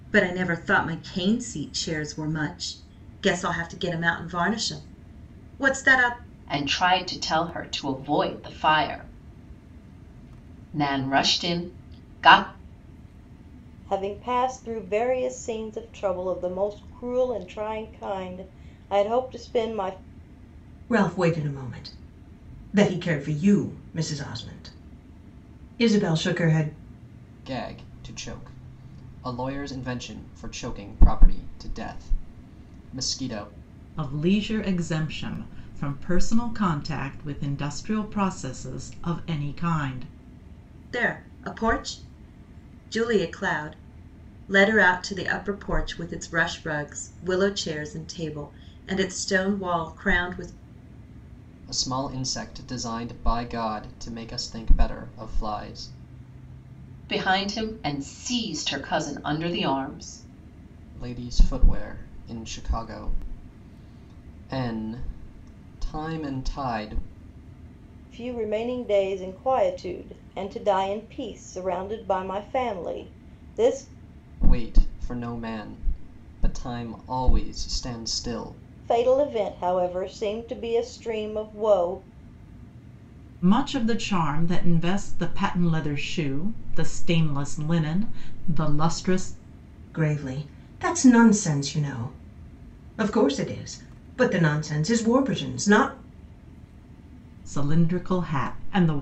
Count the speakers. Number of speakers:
6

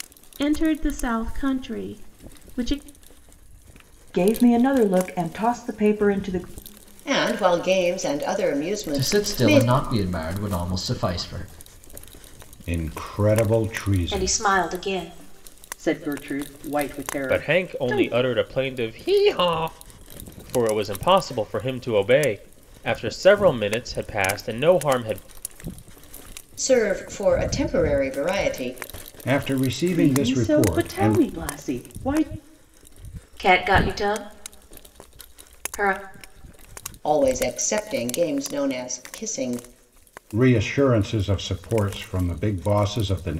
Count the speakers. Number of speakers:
8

